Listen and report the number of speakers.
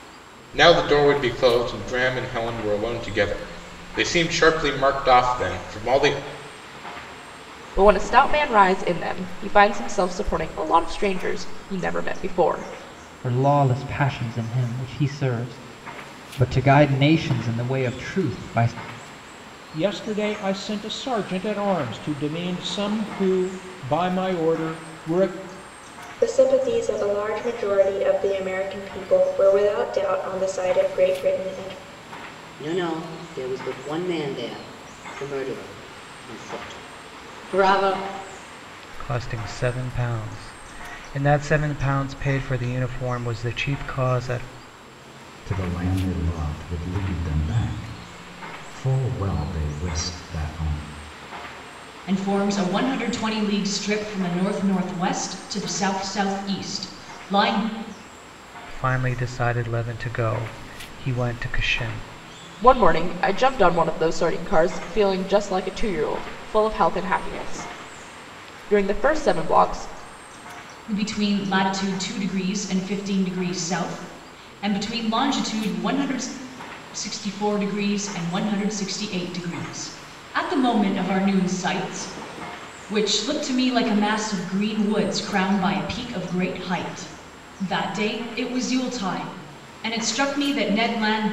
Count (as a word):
nine